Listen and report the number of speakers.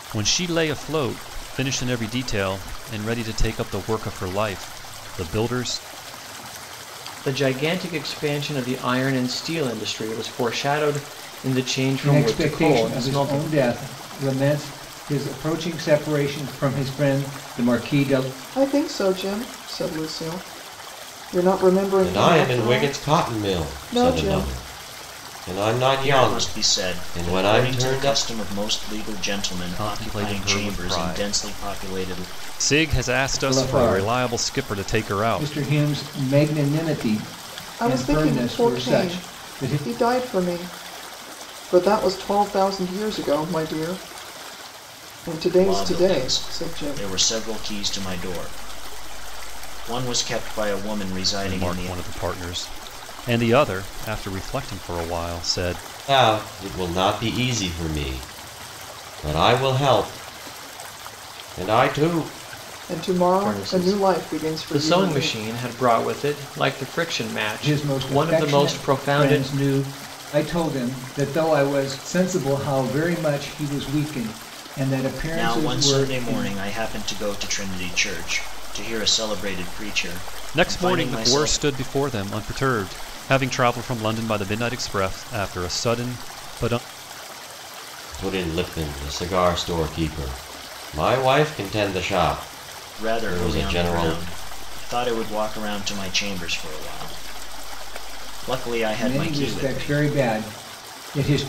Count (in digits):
6